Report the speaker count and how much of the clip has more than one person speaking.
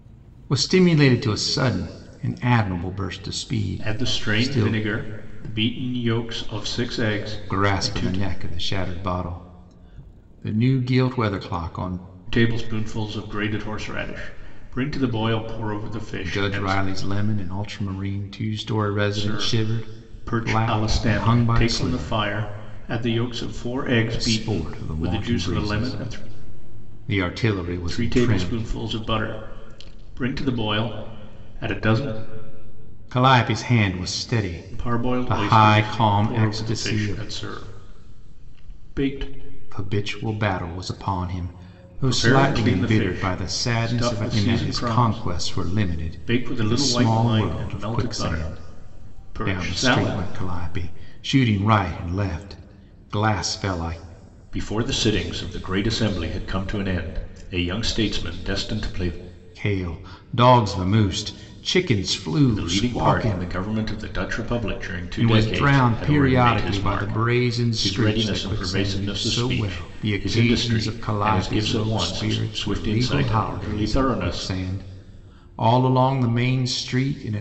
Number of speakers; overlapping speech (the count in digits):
2, about 35%